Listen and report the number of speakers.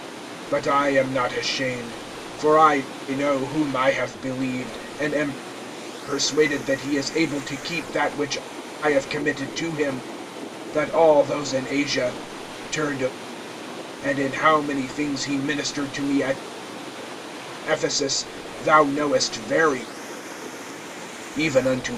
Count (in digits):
1